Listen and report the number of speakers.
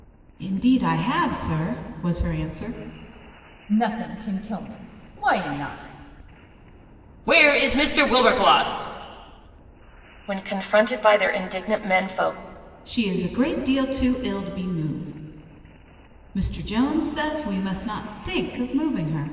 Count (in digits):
4